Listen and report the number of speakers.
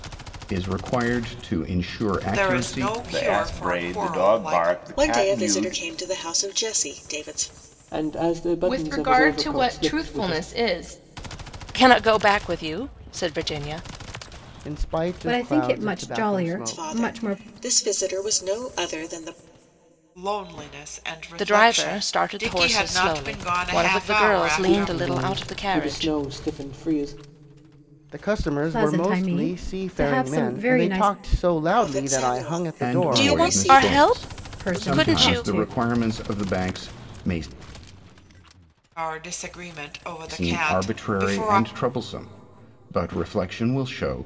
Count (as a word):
nine